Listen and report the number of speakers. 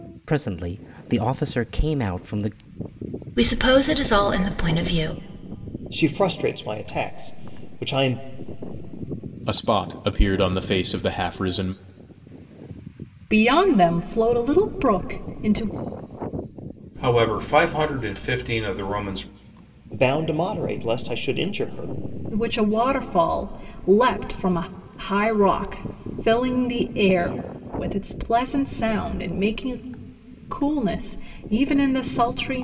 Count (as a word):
six